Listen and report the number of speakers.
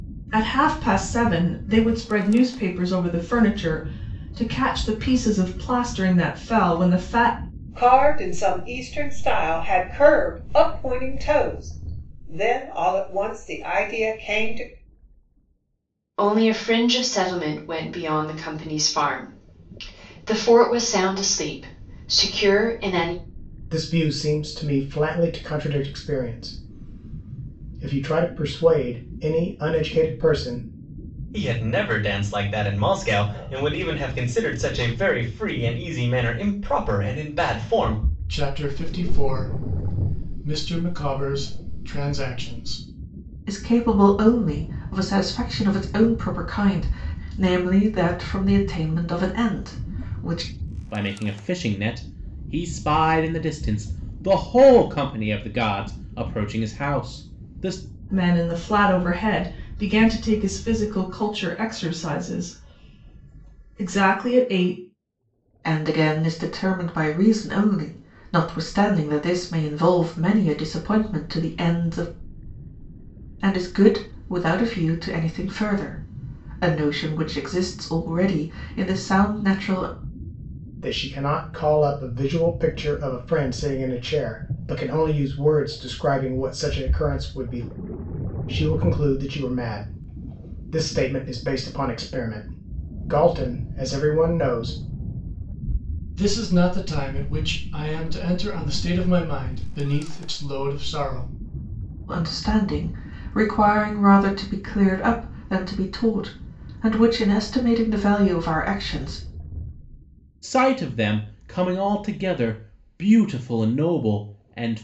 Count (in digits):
8